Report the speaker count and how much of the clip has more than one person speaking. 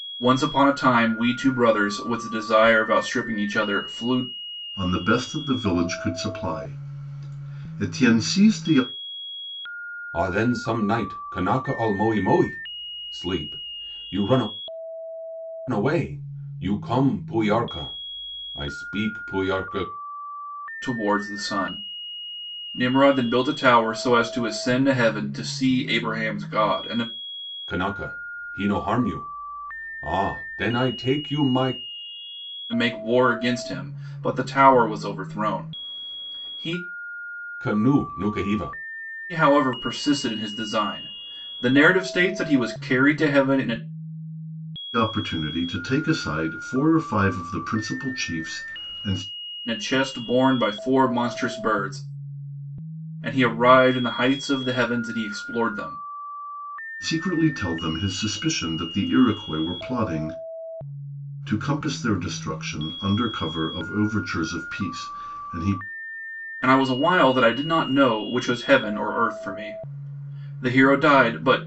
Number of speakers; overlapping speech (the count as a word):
three, no overlap